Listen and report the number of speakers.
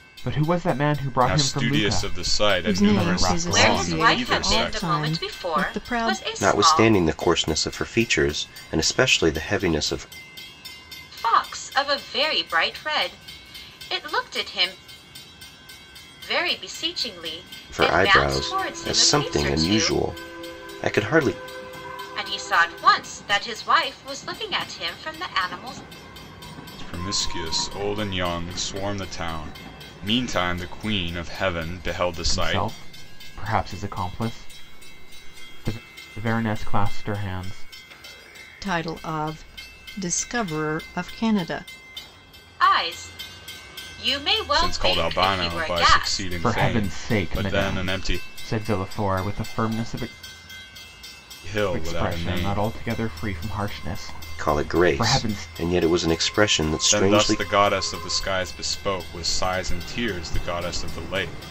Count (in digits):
5